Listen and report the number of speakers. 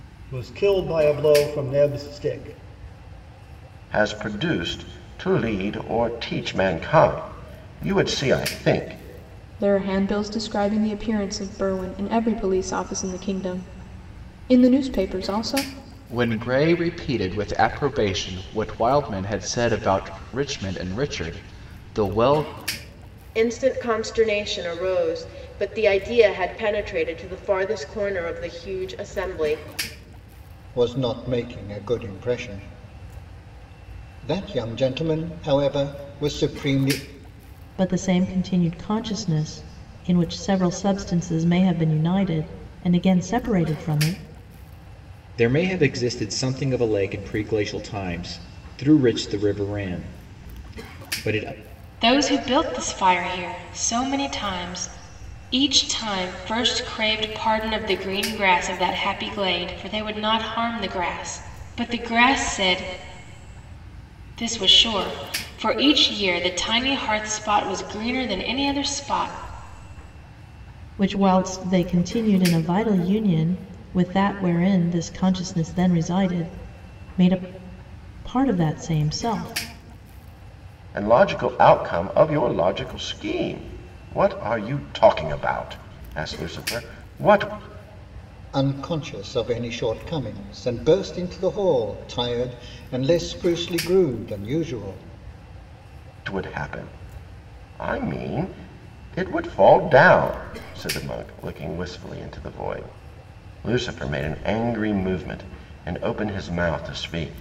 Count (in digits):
9